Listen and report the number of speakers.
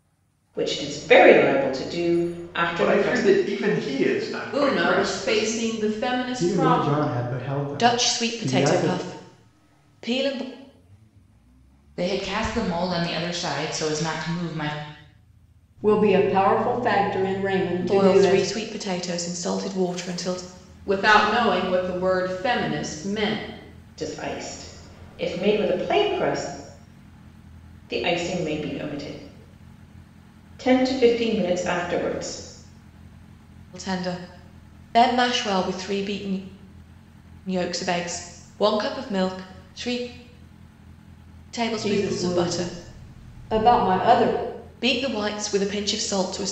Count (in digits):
7